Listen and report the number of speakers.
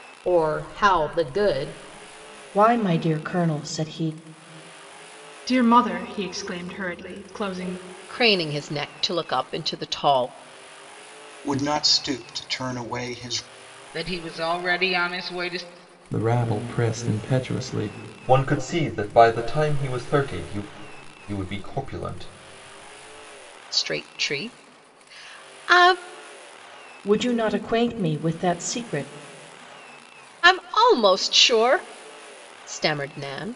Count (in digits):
8